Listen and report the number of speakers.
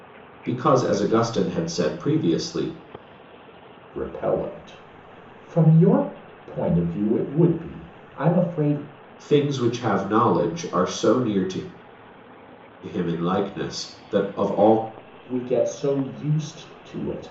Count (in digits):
2